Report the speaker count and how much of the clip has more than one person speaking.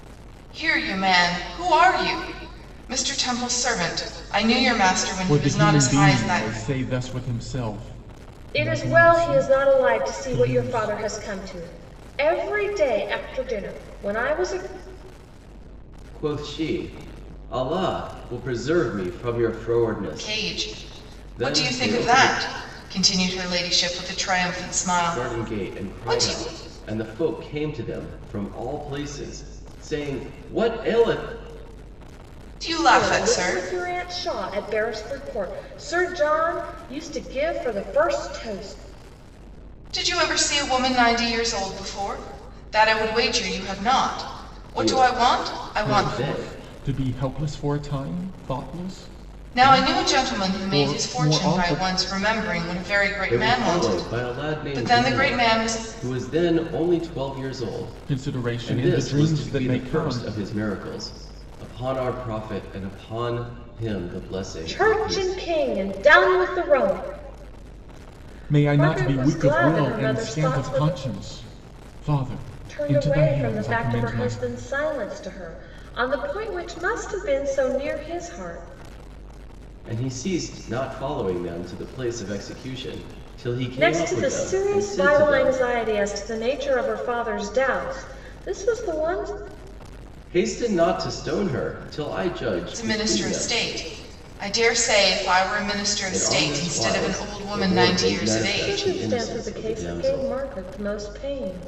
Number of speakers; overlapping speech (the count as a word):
four, about 29%